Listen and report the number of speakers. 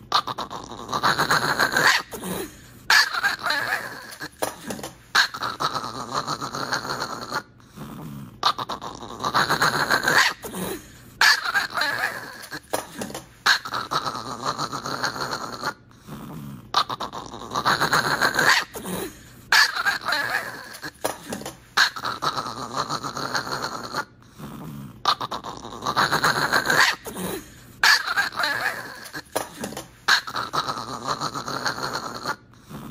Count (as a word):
zero